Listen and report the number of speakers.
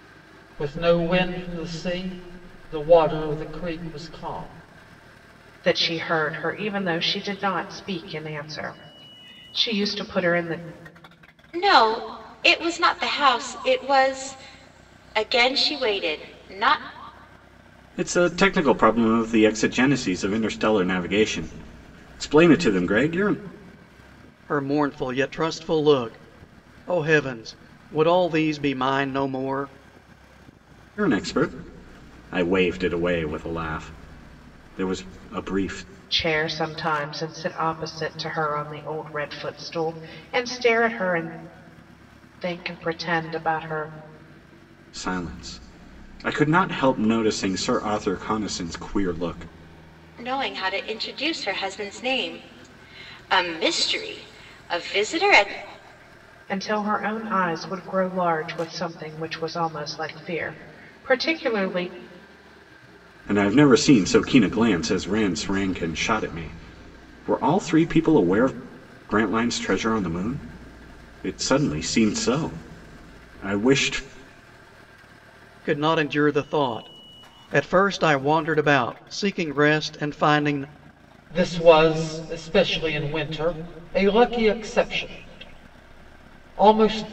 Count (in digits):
5